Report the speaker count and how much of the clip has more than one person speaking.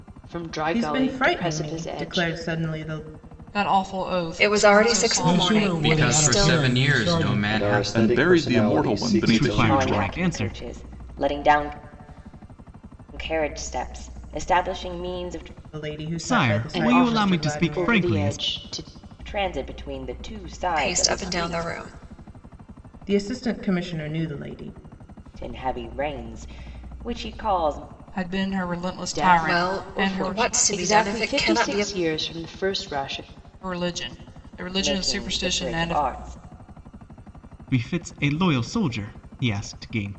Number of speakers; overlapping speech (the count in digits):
10, about 38%